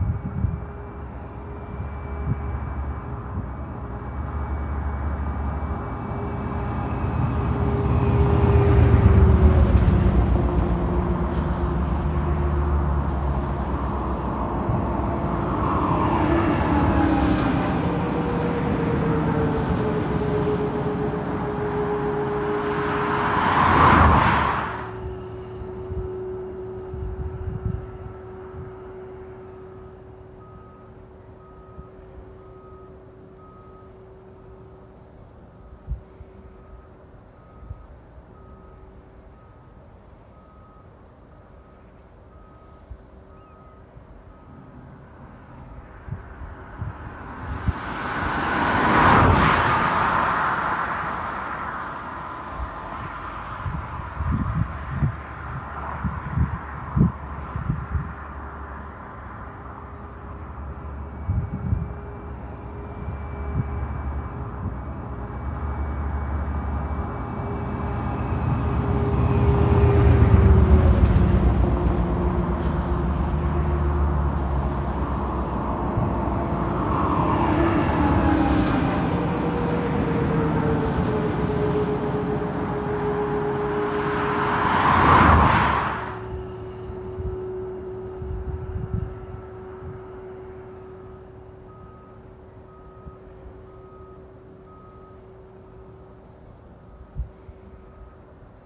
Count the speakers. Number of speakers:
zero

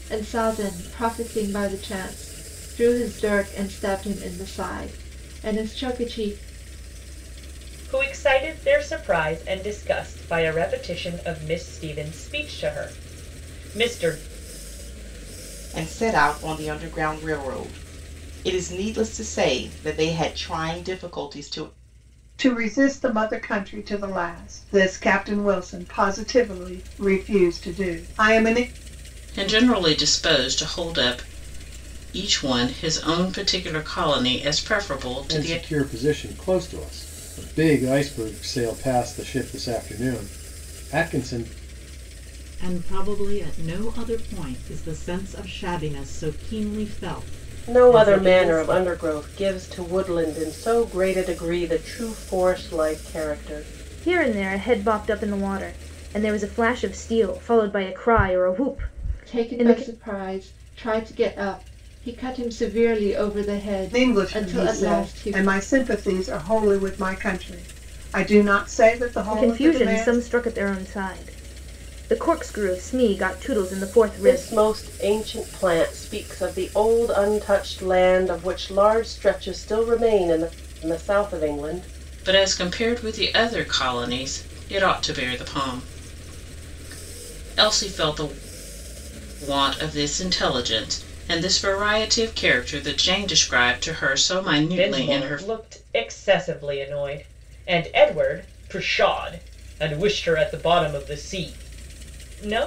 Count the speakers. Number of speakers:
nine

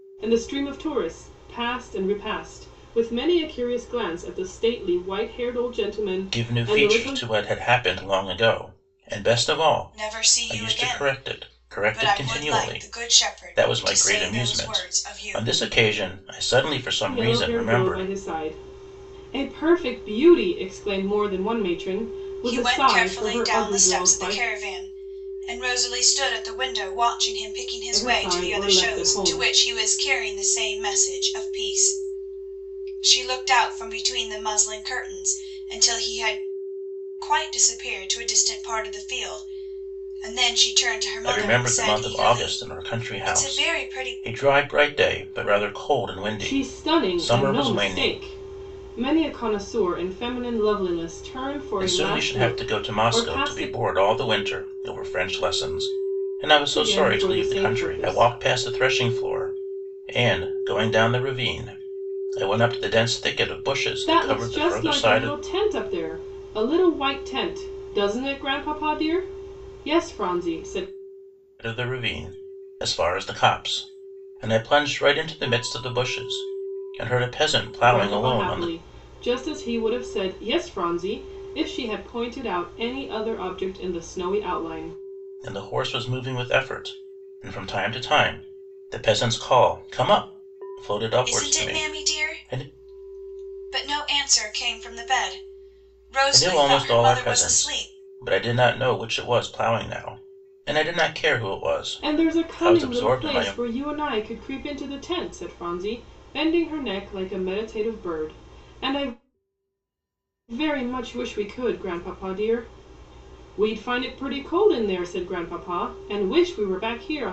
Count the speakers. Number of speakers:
three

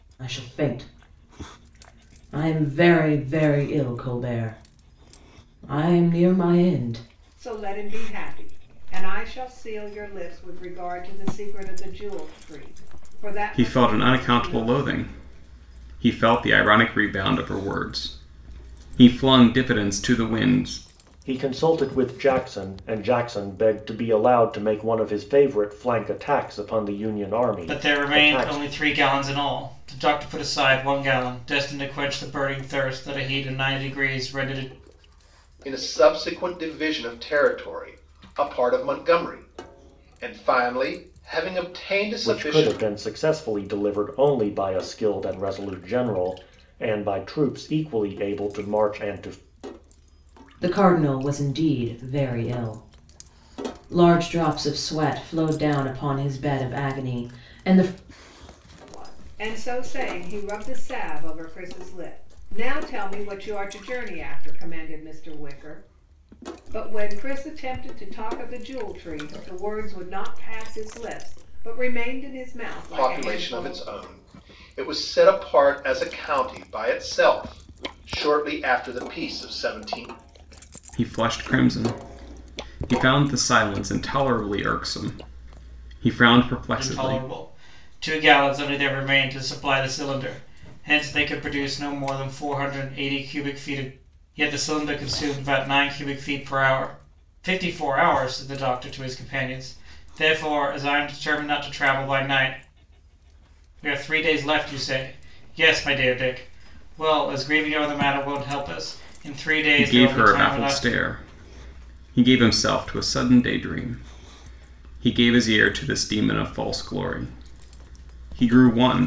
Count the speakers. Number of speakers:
six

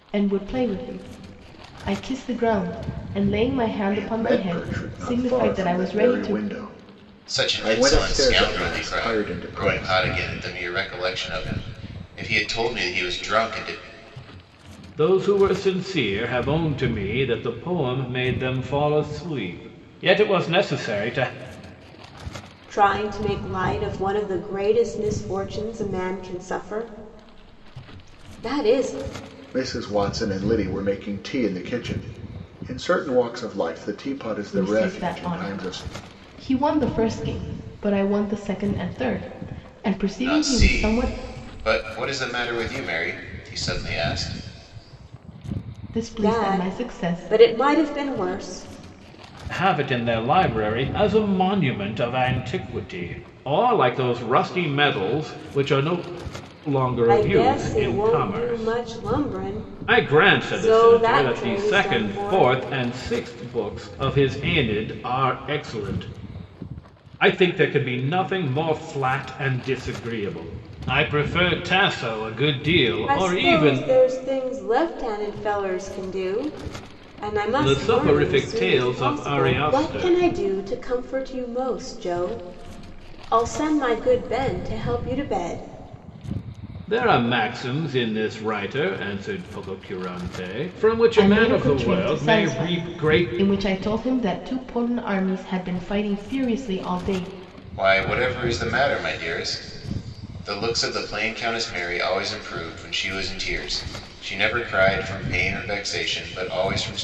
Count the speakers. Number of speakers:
five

